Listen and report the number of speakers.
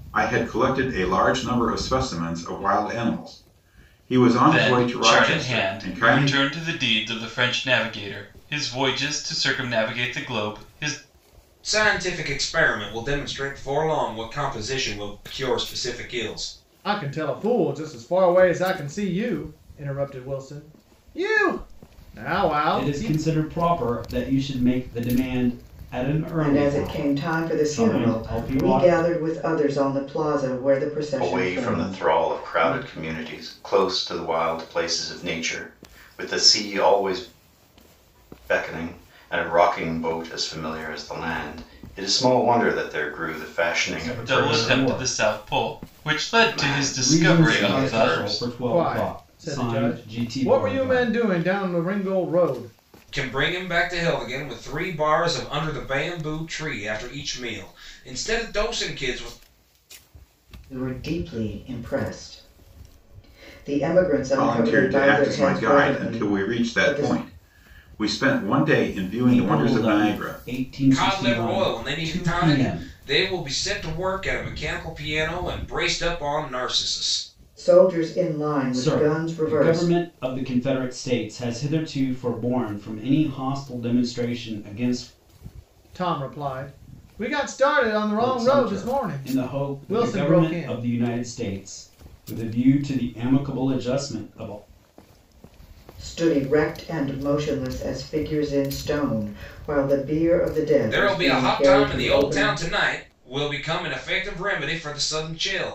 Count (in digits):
7